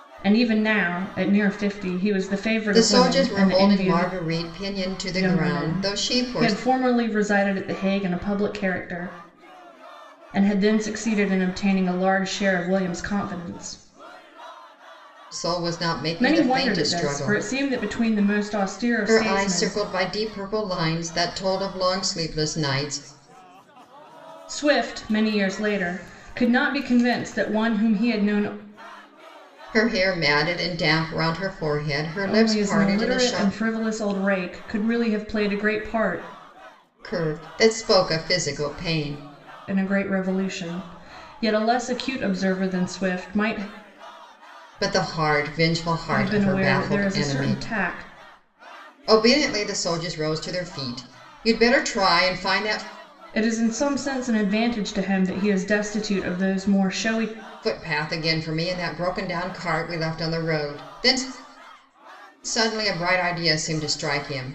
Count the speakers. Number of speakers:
2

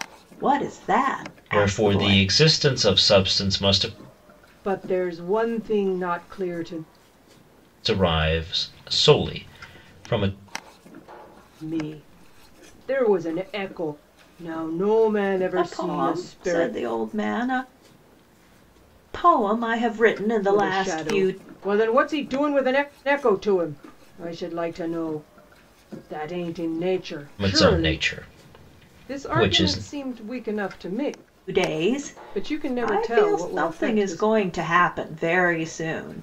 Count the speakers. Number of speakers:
3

